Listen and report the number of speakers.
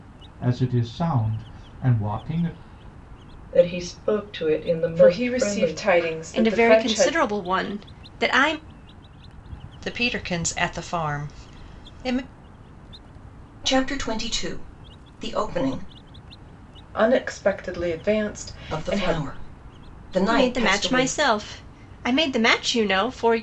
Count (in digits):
6